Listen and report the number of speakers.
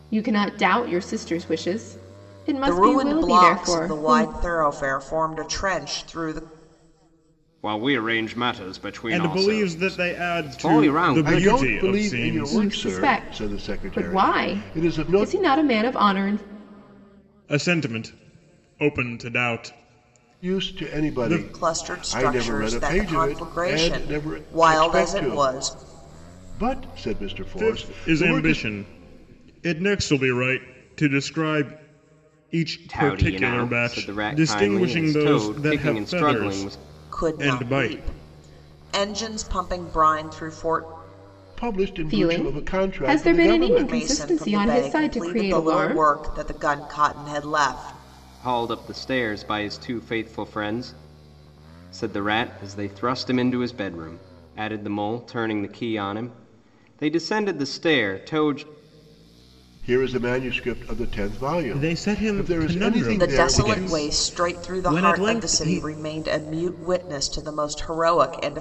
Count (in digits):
5